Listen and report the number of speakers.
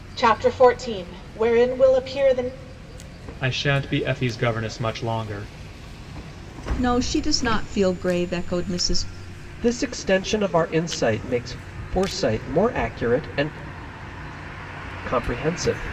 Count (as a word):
four